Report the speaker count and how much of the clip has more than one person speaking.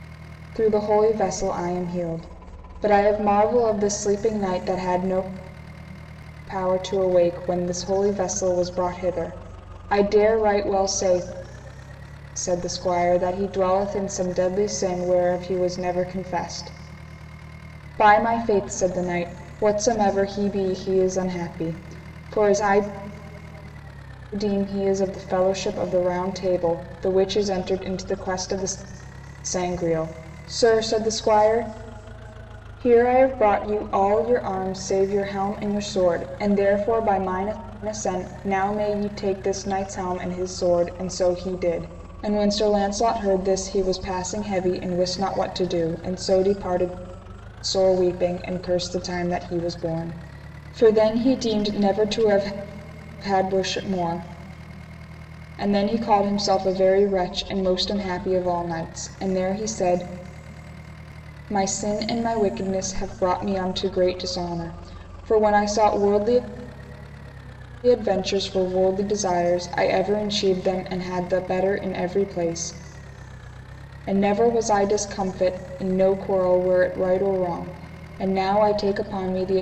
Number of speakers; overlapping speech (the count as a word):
one, no overlap